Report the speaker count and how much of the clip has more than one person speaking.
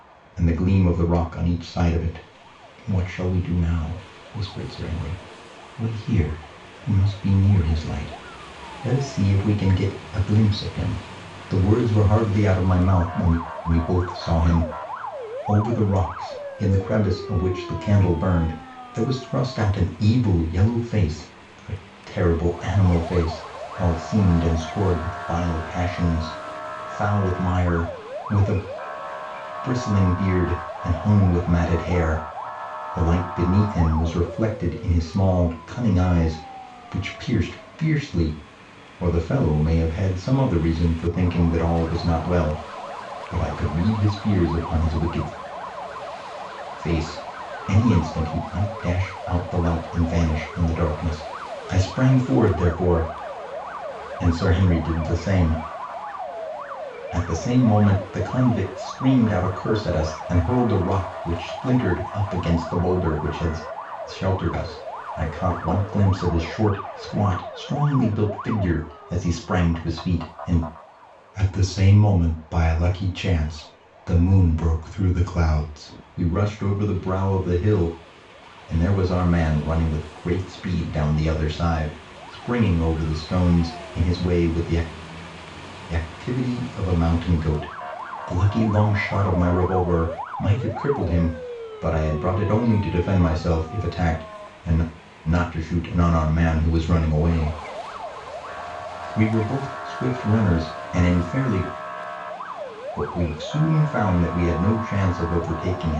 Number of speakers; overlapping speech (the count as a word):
one, no overlap